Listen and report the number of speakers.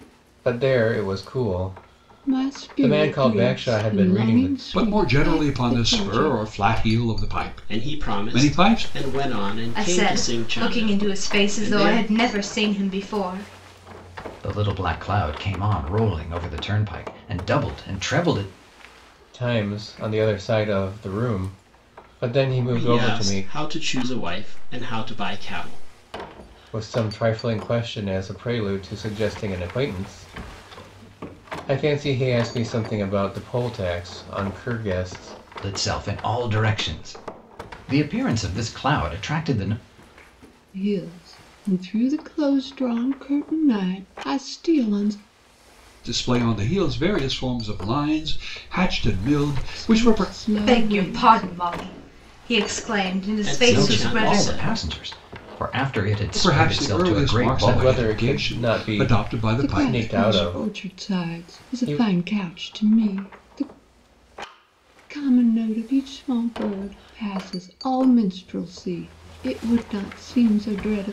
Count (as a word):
six